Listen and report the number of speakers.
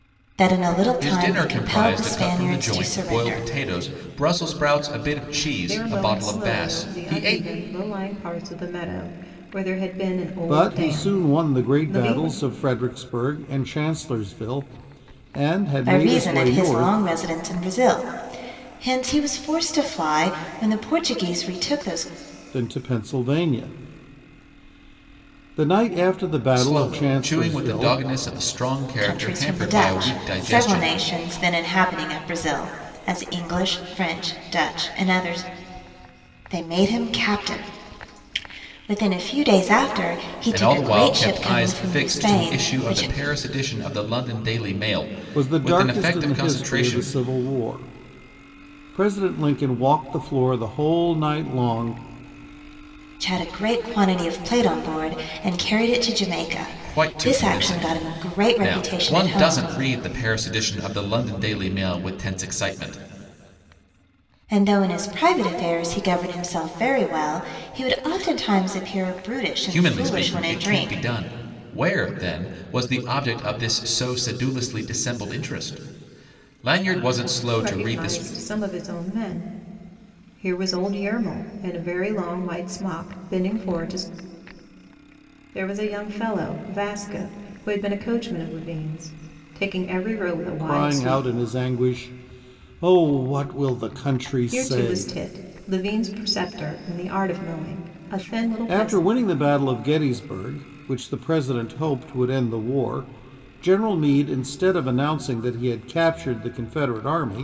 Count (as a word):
four